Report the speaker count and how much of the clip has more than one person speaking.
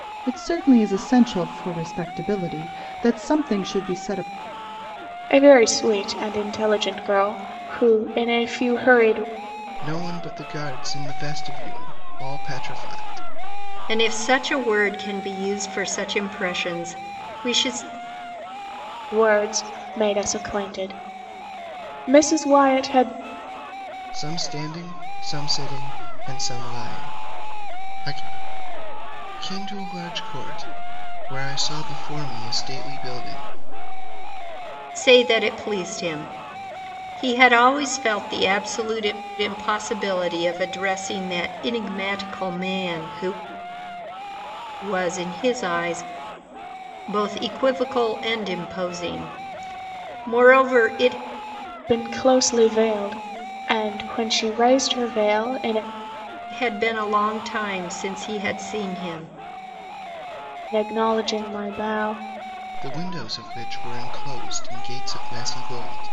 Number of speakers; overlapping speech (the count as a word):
four, no overlap